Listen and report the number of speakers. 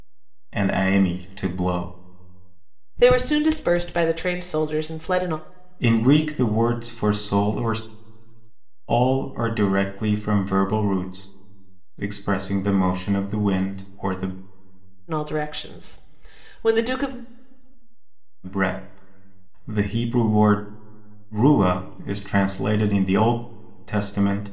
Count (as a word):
two